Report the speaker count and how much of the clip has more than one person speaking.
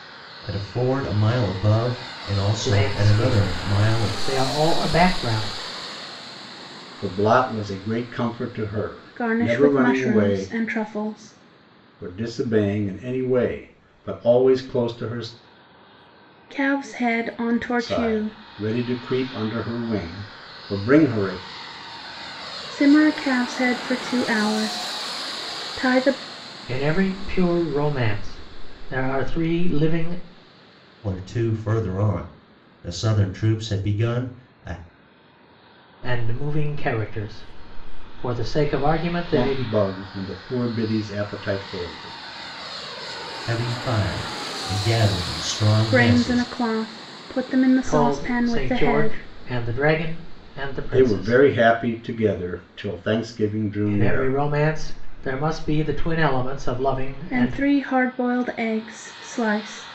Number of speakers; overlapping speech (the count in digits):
4, about 12%